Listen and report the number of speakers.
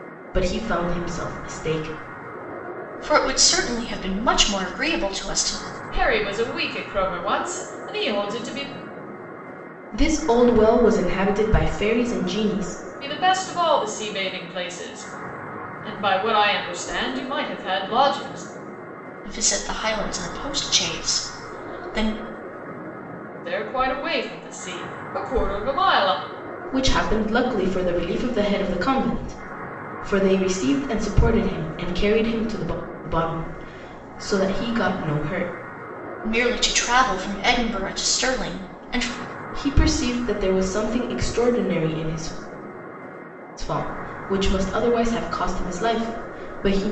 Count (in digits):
3